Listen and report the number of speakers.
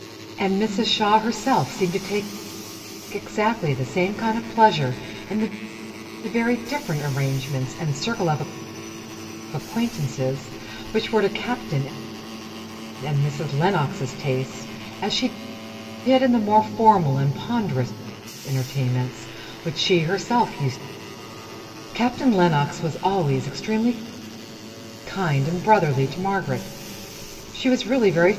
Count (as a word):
one